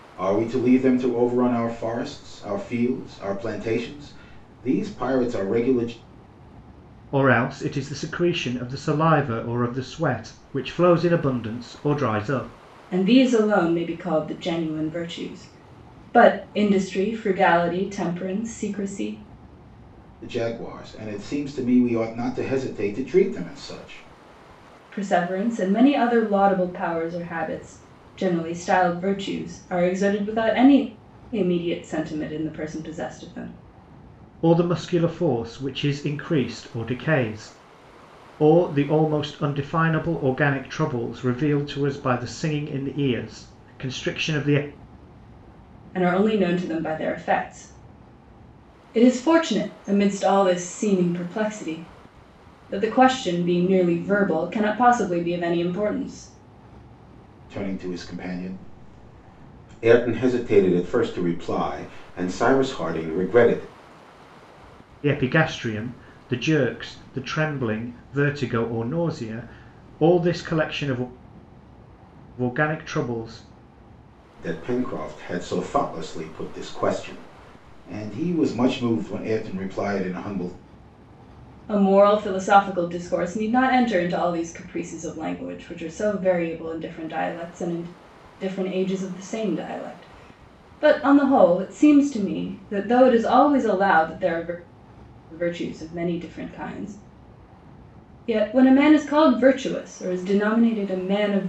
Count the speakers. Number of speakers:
three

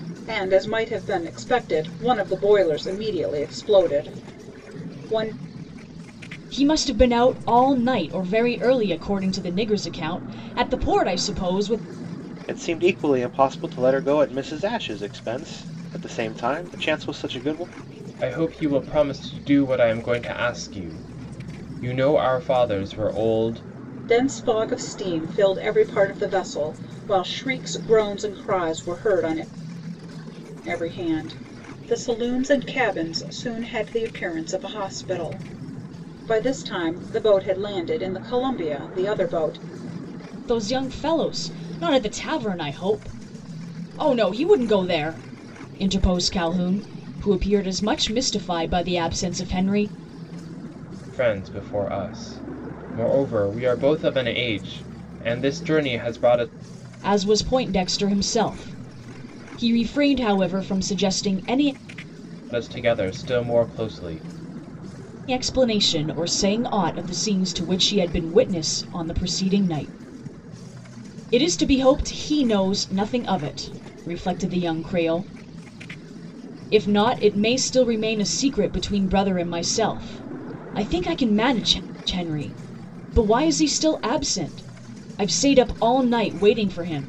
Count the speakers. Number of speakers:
four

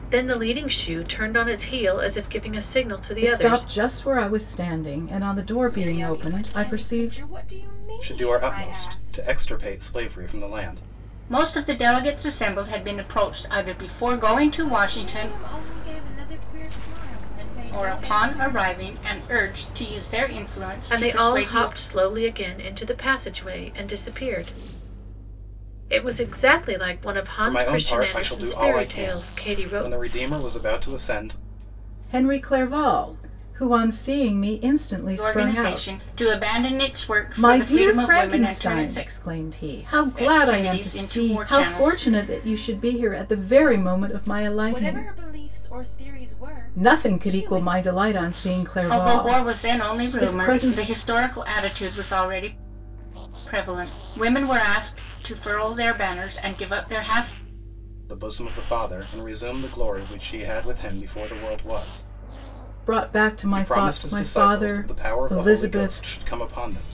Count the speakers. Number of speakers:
five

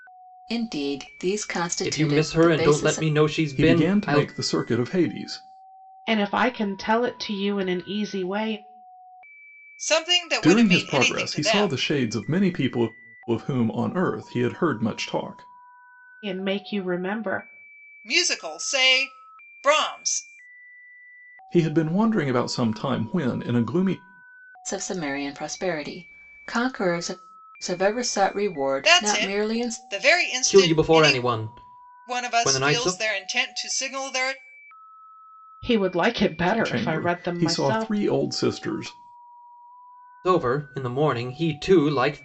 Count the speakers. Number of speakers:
five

